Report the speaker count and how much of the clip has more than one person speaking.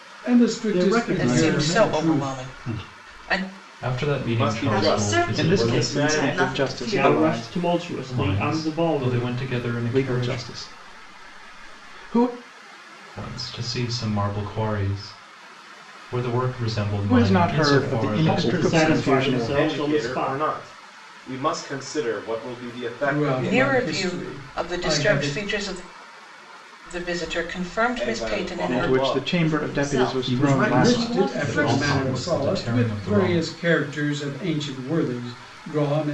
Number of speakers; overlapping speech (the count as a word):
eight, about 51%